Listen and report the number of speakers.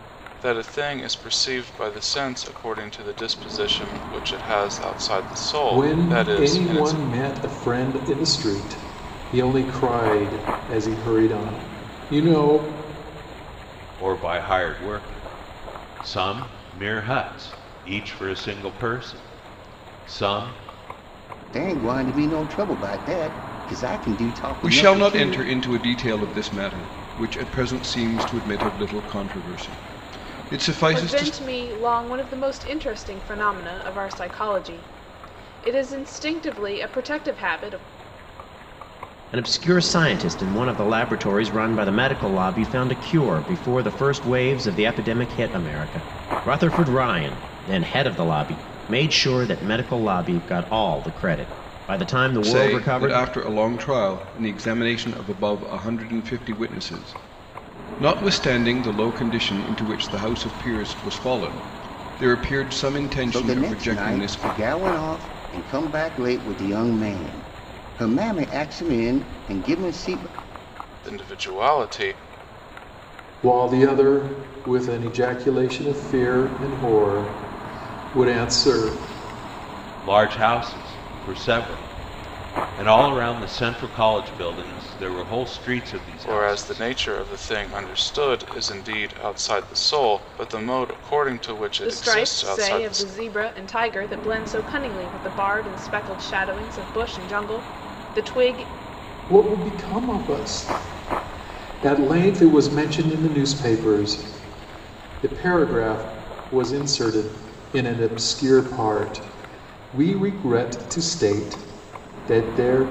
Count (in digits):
7